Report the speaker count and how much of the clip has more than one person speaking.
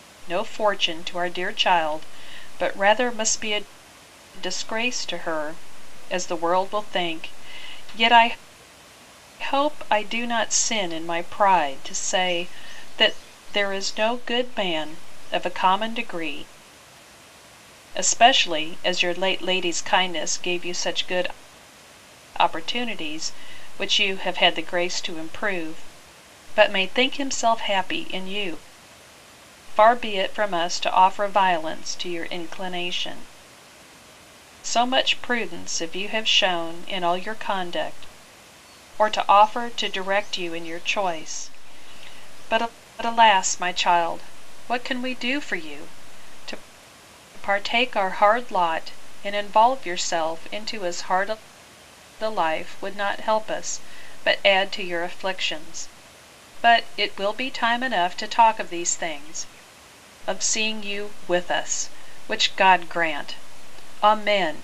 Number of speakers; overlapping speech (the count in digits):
1, no overlap